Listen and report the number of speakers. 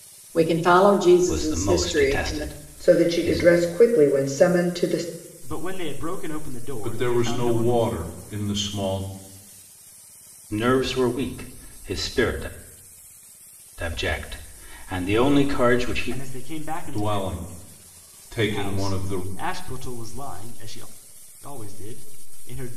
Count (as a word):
five